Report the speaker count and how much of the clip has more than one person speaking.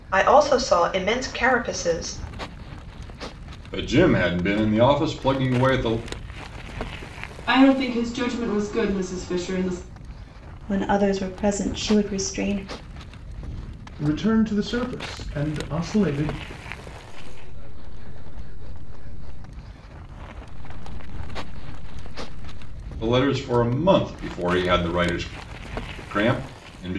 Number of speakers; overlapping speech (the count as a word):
six, no overlap